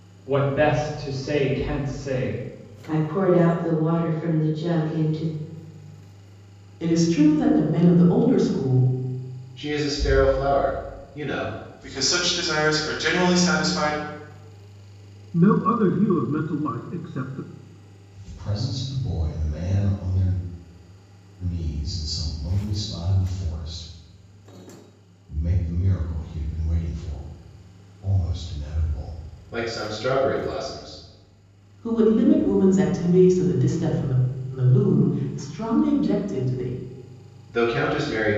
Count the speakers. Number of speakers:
seven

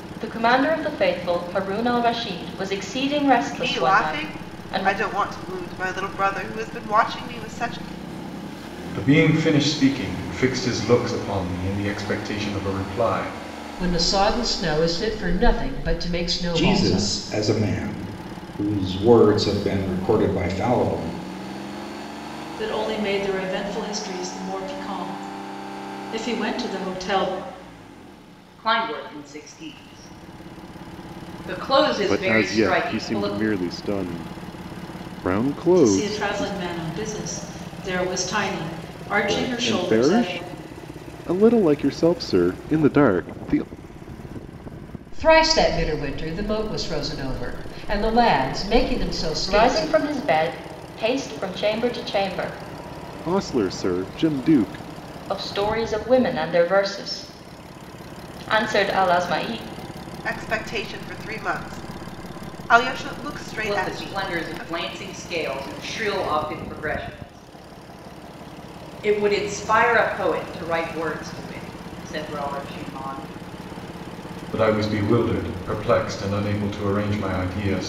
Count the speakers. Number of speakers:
eight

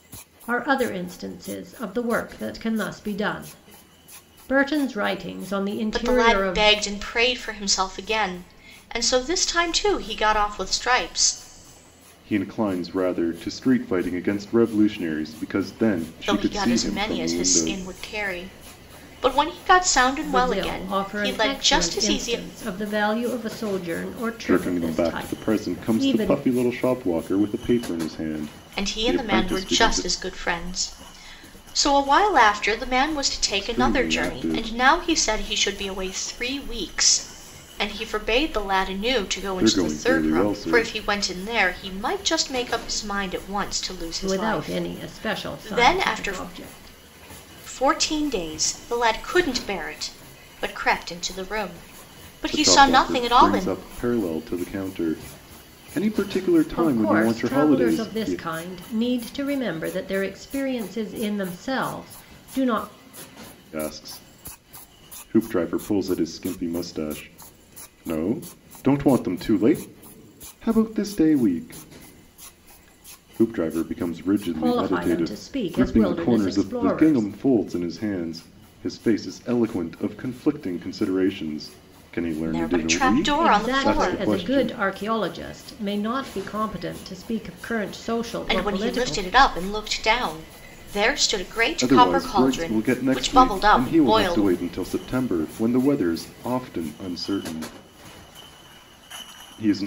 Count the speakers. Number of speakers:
three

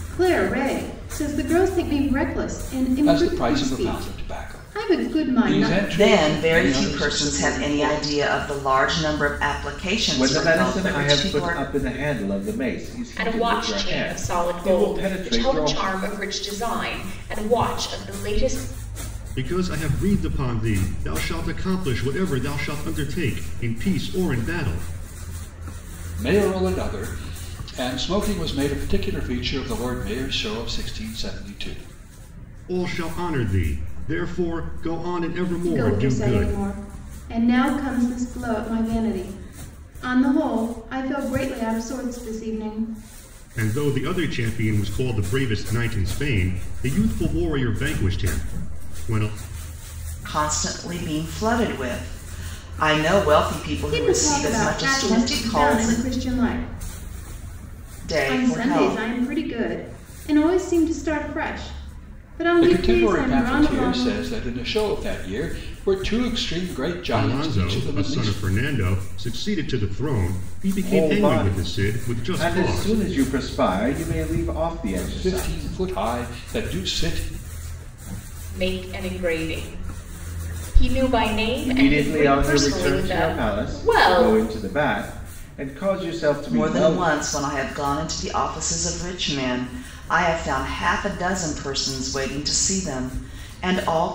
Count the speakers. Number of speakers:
six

